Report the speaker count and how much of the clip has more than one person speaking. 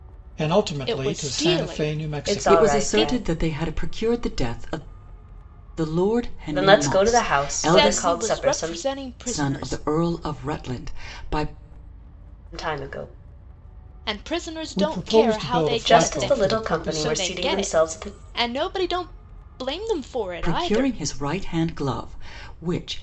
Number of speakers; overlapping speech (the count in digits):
4, about 41%